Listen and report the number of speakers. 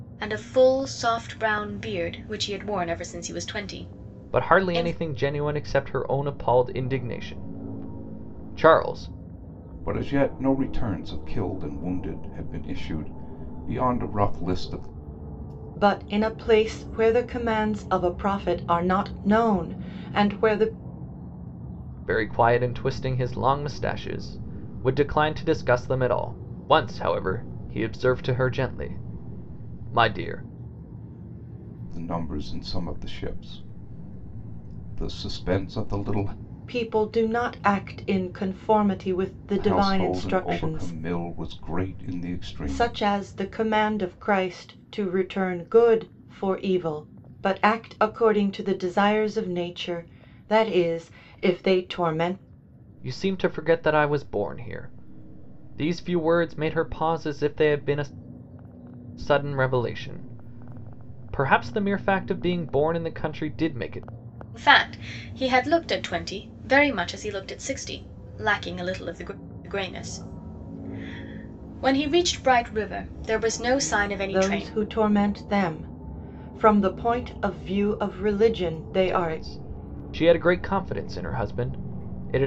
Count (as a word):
four